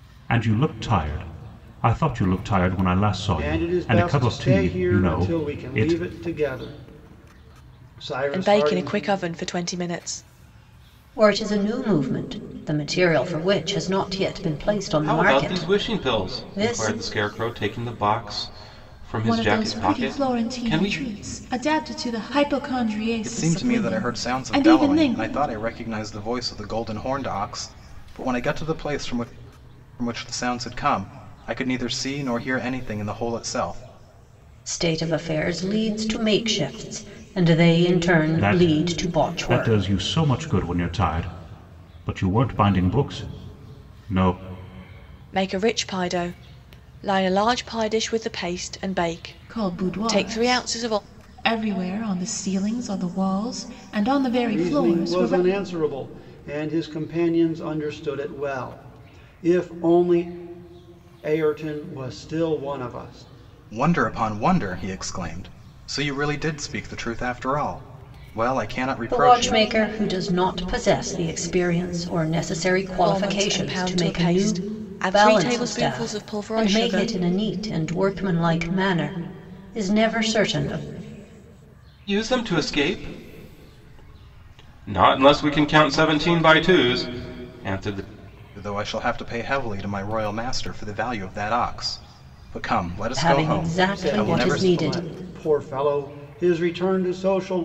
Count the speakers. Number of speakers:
seven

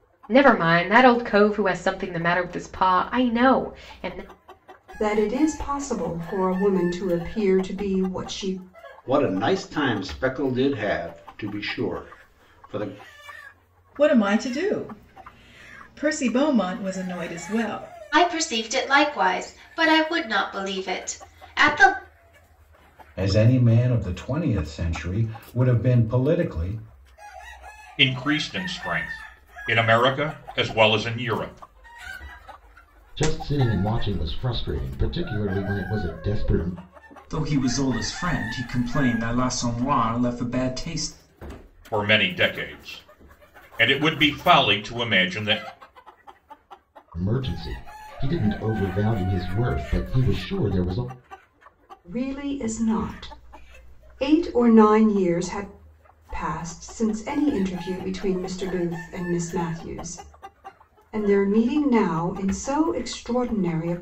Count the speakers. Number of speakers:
nine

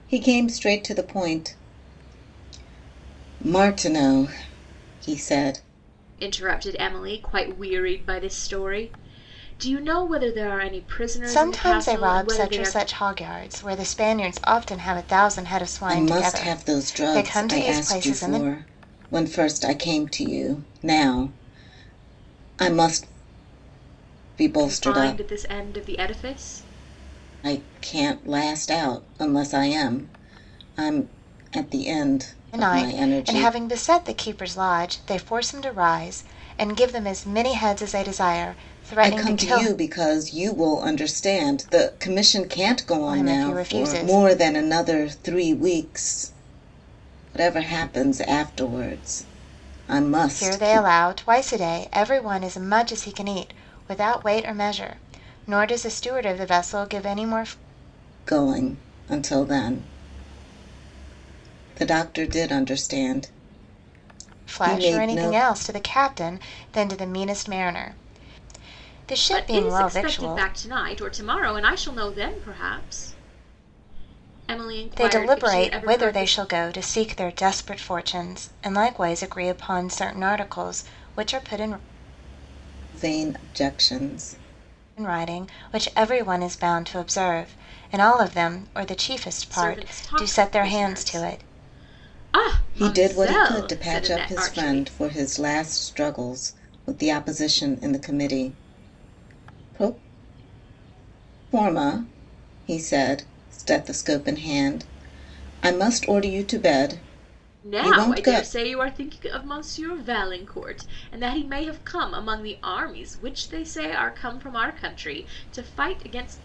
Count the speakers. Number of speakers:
three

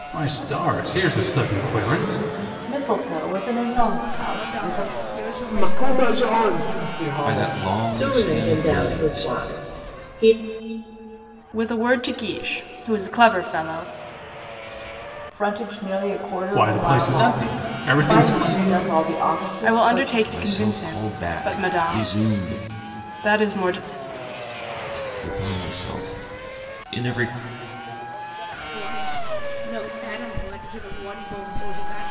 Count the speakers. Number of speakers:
seven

